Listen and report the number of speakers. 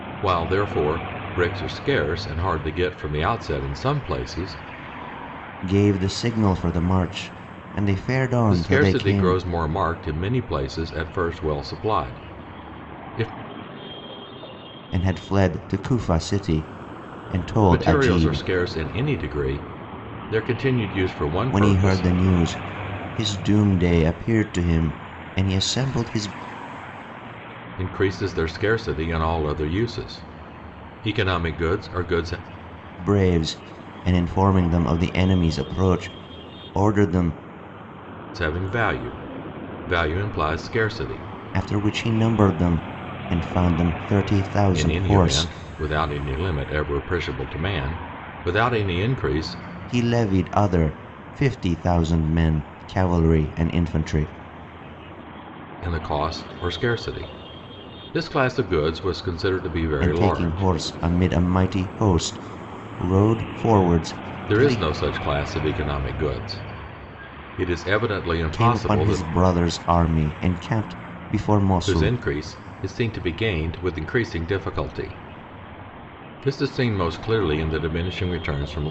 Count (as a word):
two